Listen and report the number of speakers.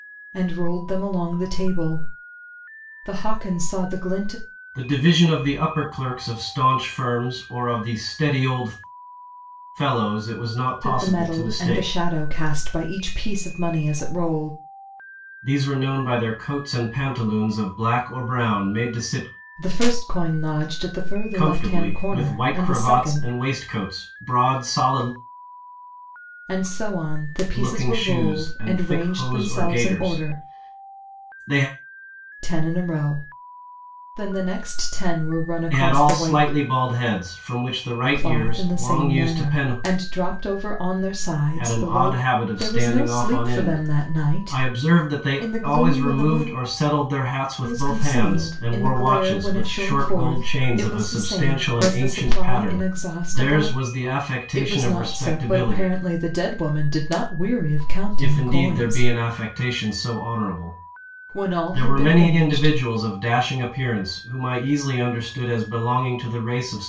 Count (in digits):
2